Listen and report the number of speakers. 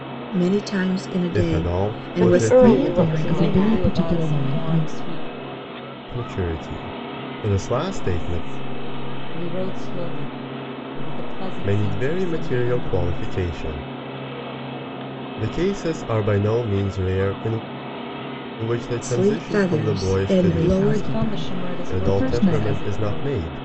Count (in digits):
5